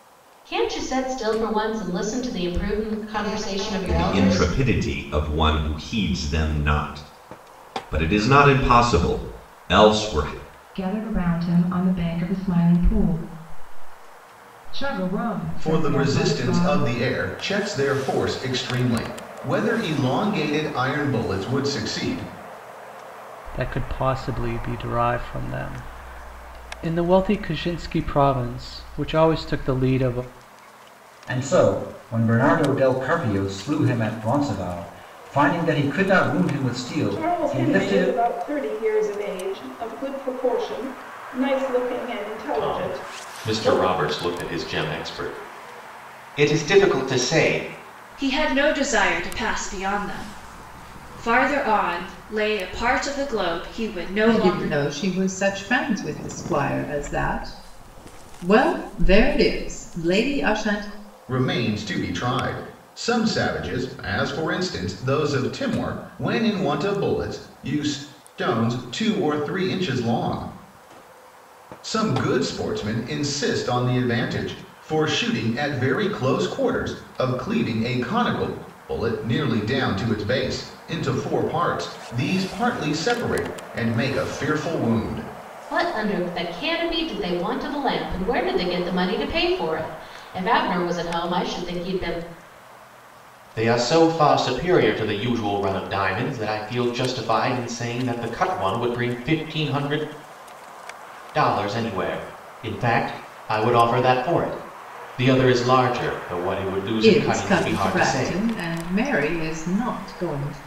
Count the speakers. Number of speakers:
10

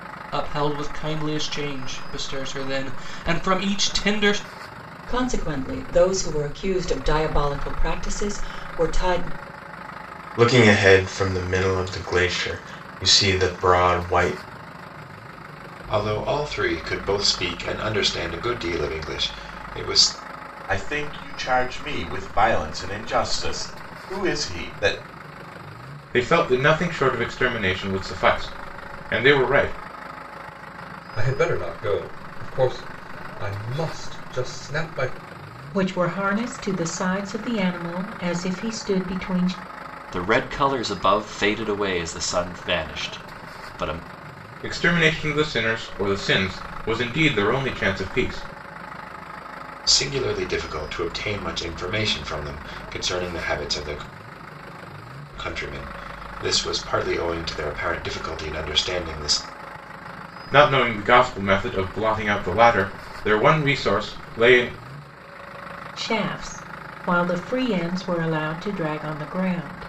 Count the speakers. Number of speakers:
9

